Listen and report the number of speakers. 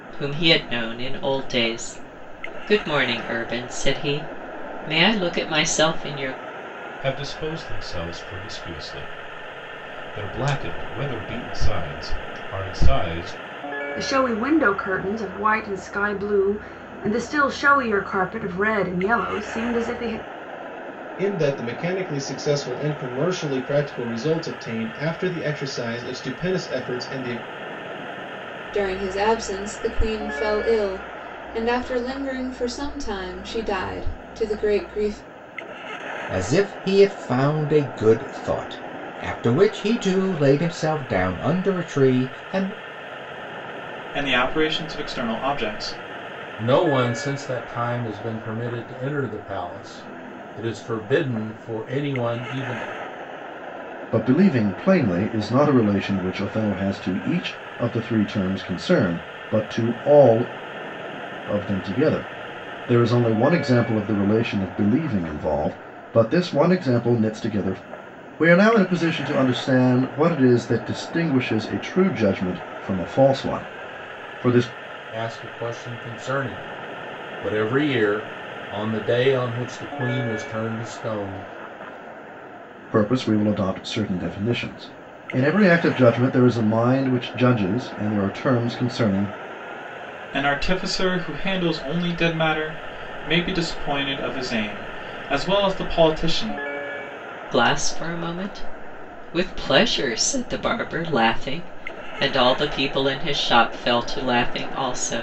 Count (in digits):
9